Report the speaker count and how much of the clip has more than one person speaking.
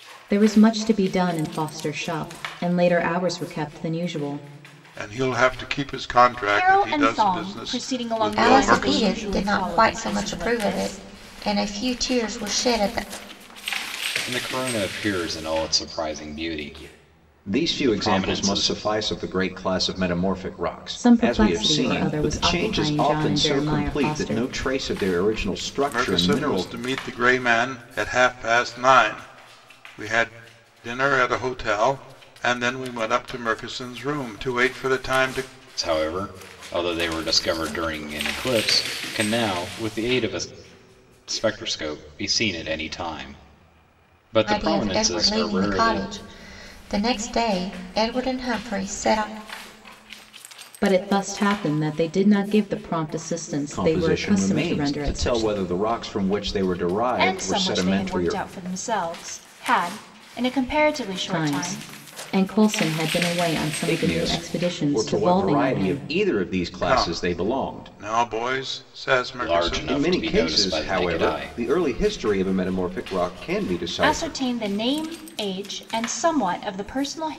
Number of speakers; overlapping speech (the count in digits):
6, about 28%